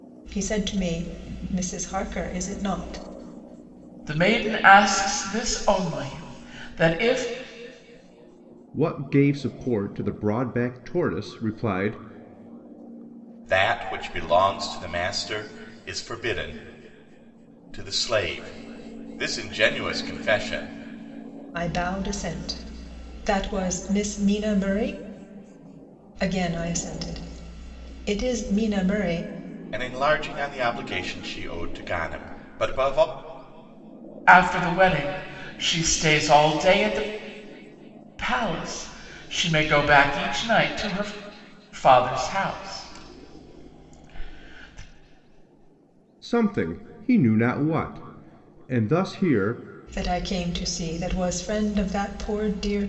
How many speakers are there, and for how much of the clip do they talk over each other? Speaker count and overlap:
four, no overlap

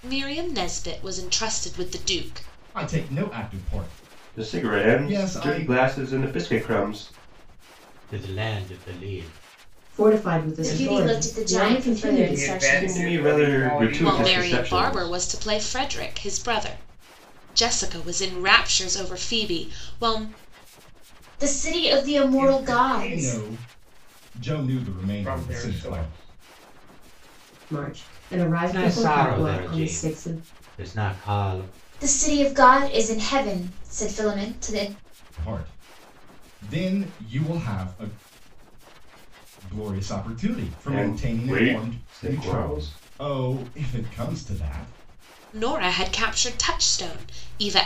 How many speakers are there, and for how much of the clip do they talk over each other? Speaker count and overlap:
seven, about 26%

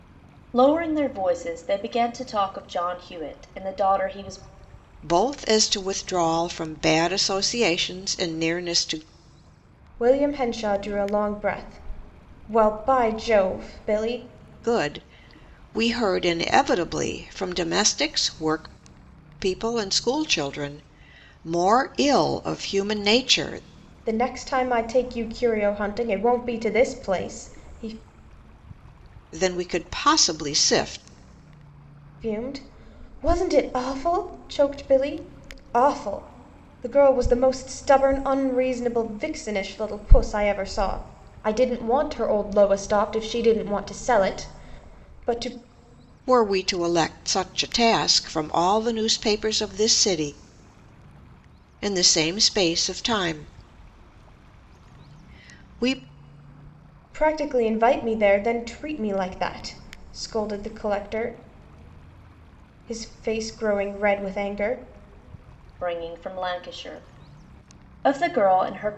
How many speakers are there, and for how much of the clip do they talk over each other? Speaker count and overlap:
three, no overlap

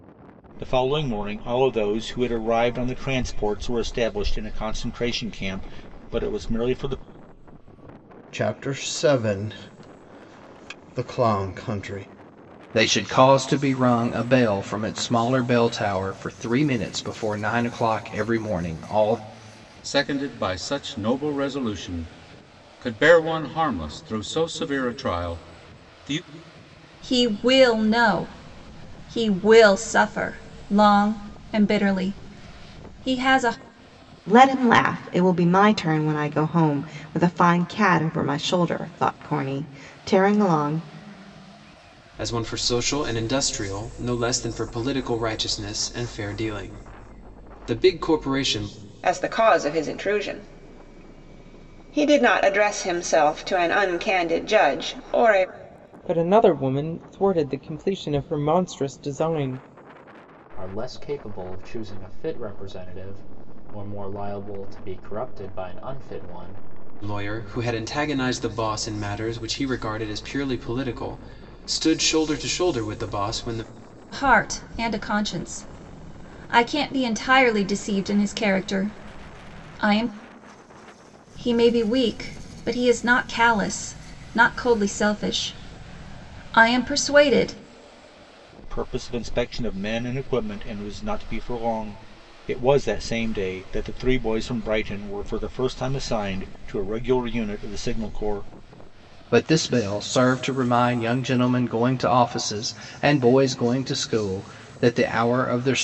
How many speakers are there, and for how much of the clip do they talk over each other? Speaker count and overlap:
ten, no overlap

